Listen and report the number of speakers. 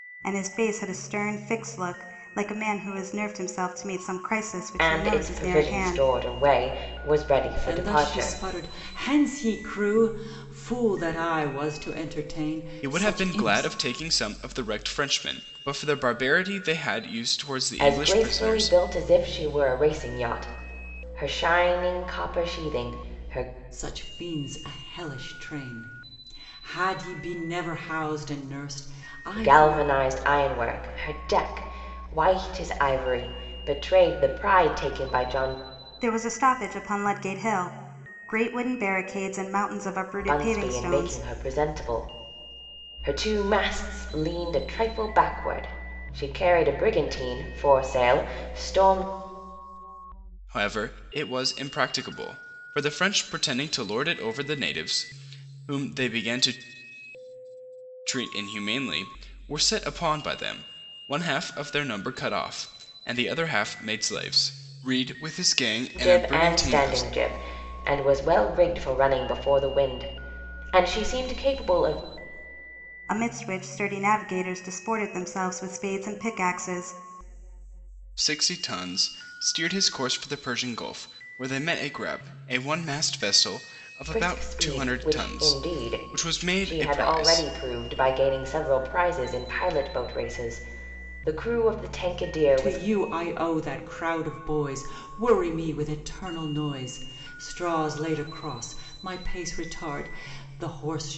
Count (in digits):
4